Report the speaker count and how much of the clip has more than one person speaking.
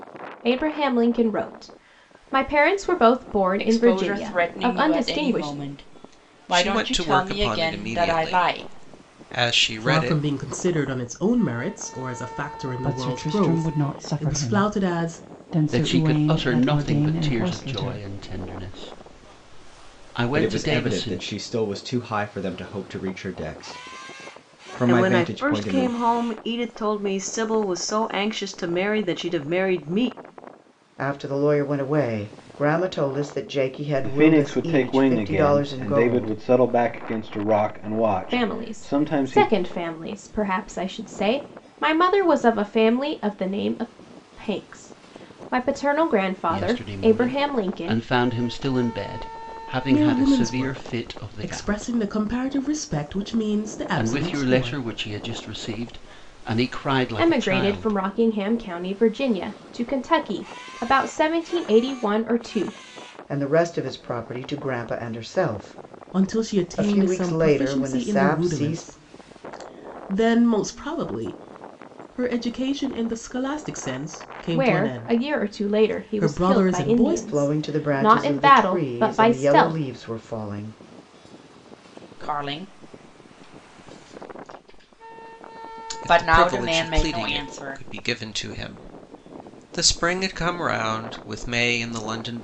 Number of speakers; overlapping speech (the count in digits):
10, about 34%